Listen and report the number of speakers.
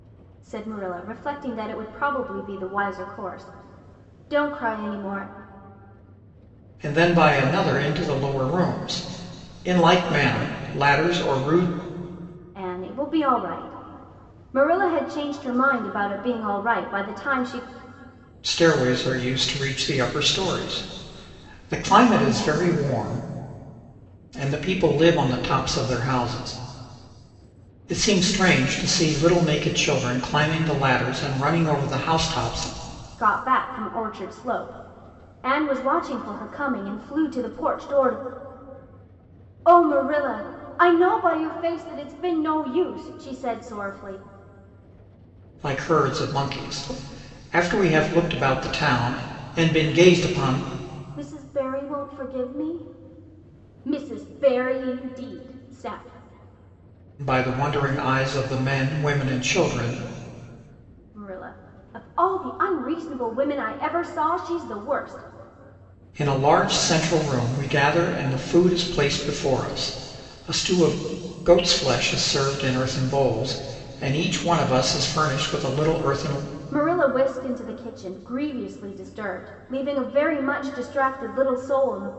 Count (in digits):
2